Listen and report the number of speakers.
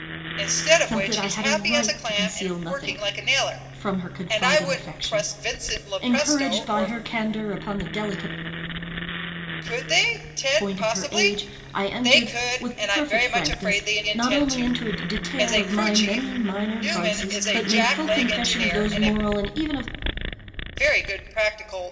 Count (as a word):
two